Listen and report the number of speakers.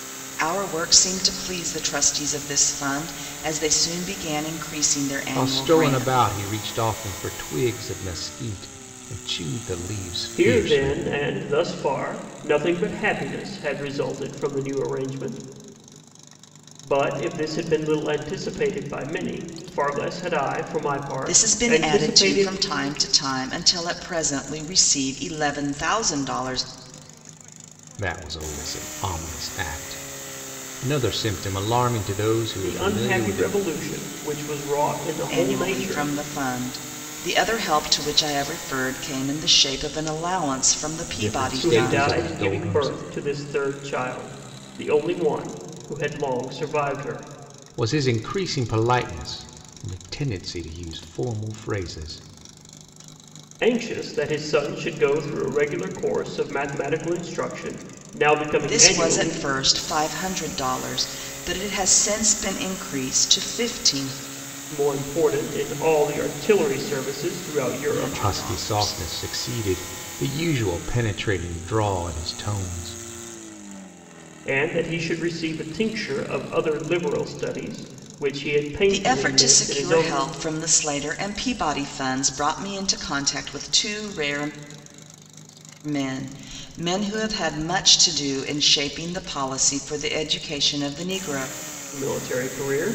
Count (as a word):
three